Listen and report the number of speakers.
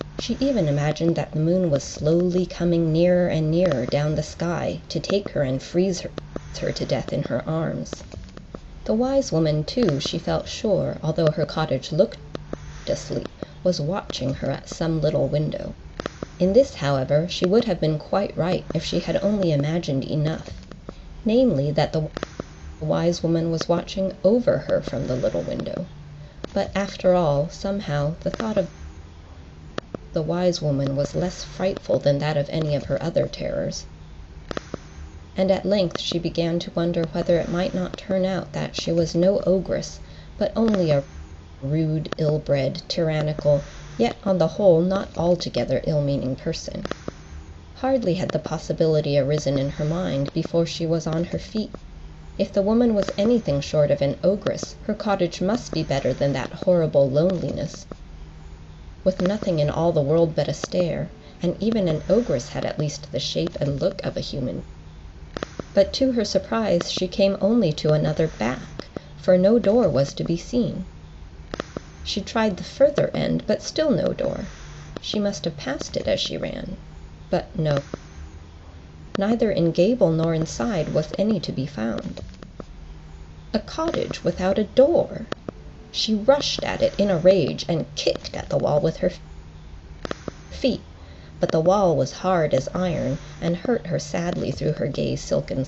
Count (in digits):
1